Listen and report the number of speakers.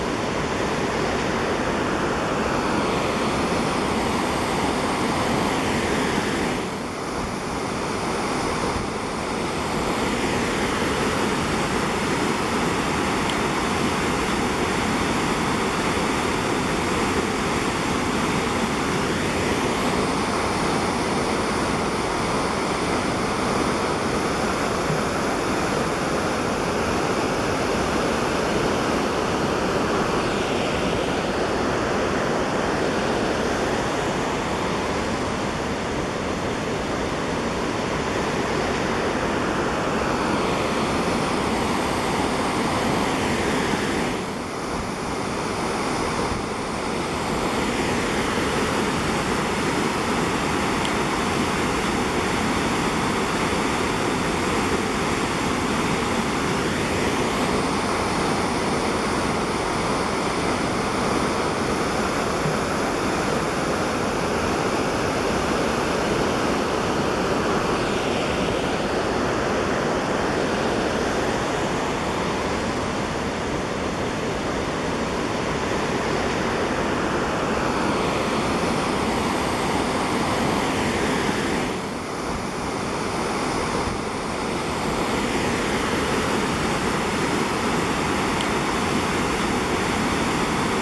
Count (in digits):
0